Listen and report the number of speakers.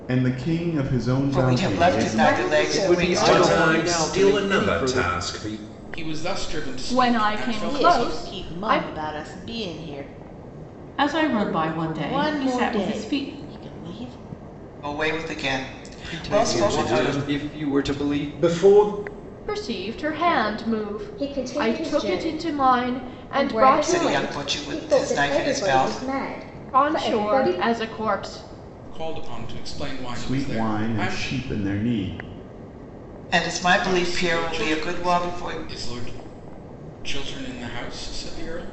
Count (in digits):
9